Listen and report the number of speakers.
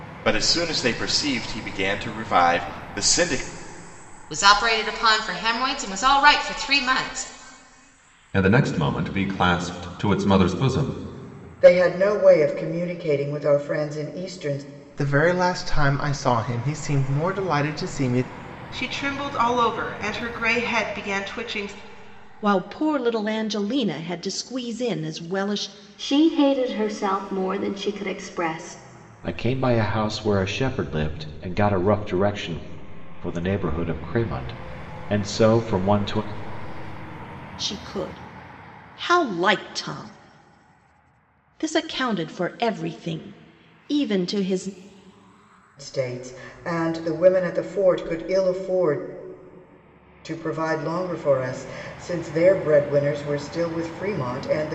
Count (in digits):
9